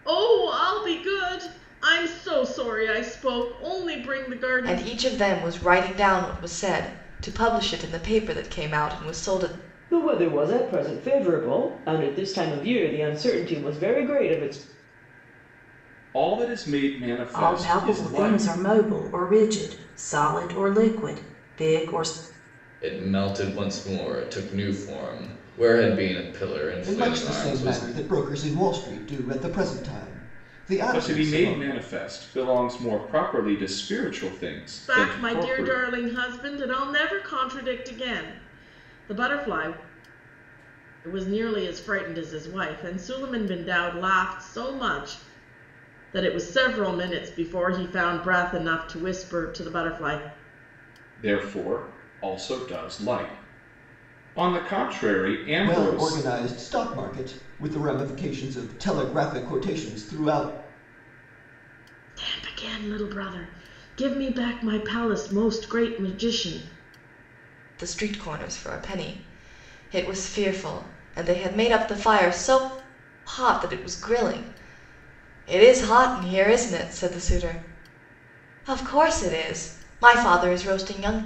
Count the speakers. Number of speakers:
seven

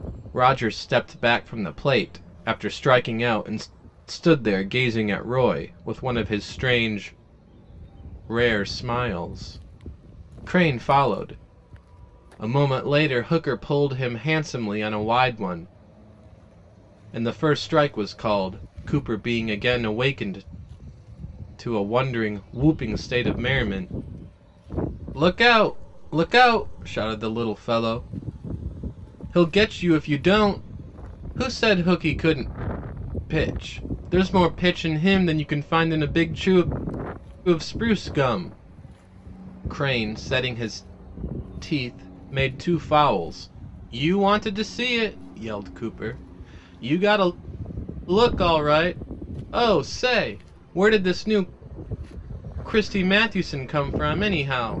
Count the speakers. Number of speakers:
one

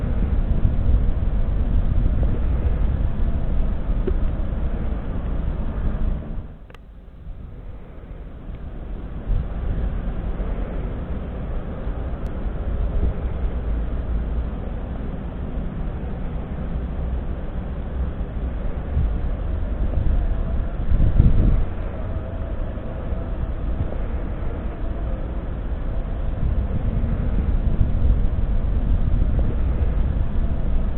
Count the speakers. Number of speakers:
zero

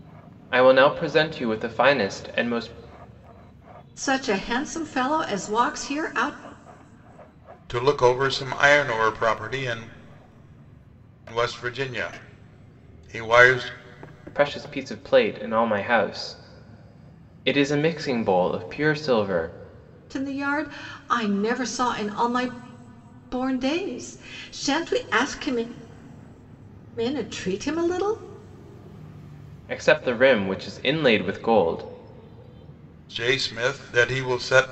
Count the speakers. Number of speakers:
three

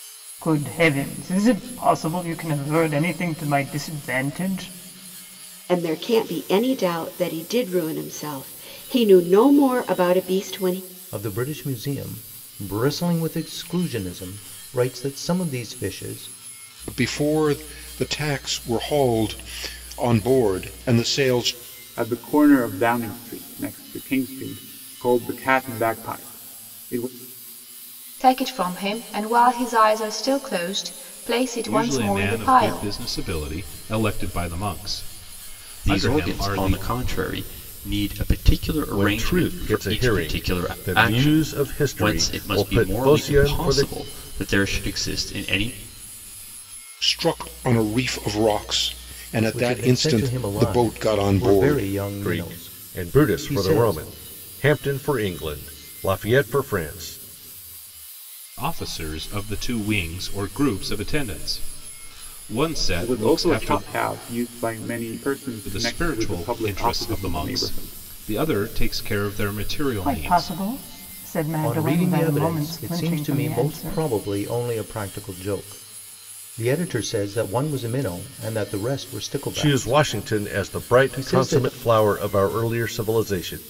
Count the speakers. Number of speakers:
nine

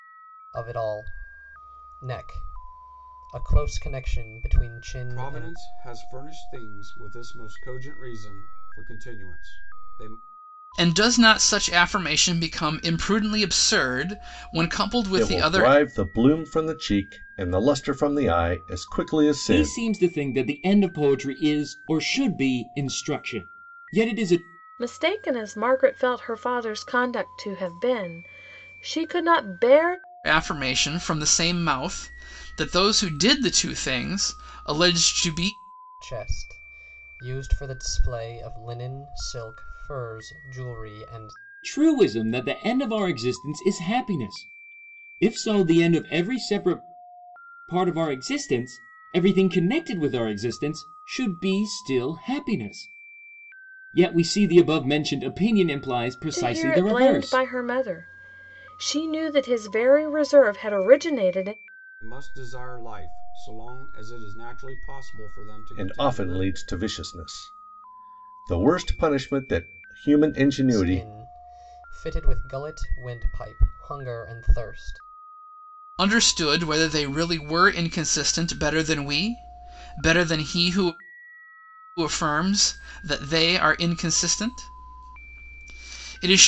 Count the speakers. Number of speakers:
six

